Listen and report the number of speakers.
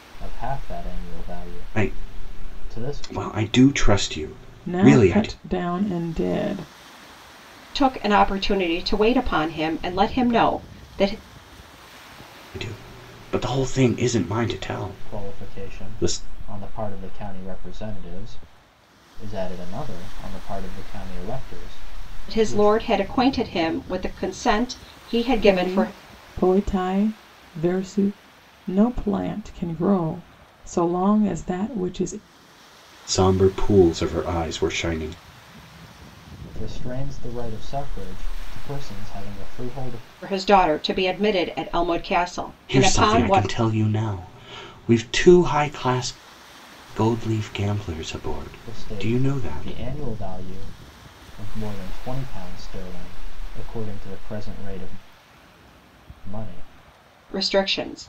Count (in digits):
4